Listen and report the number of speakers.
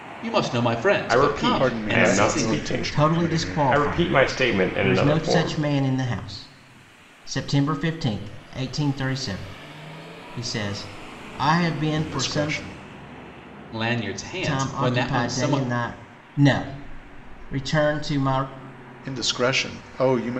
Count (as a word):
four